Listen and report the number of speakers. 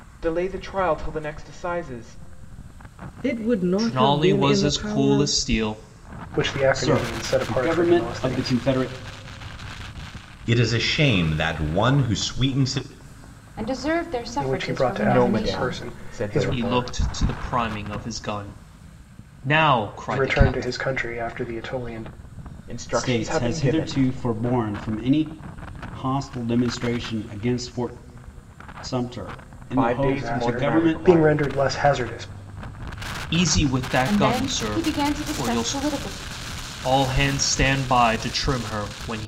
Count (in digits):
7